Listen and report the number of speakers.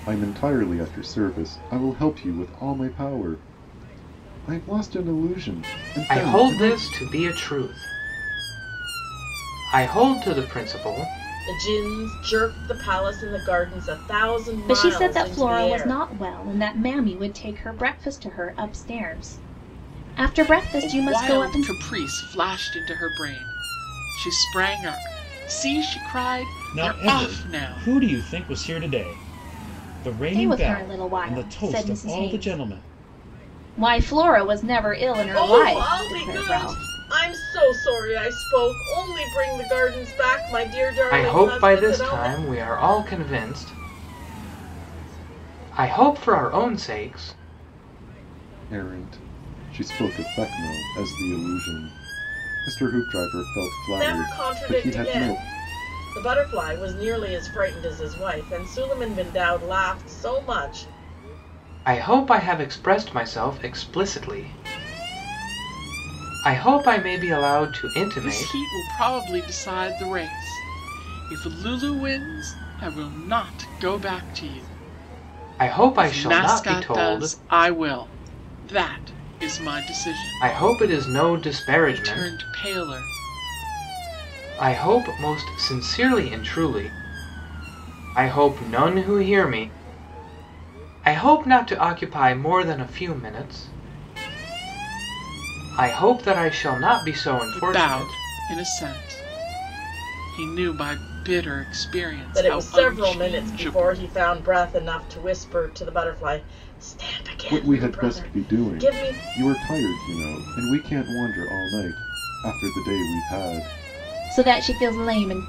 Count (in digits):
6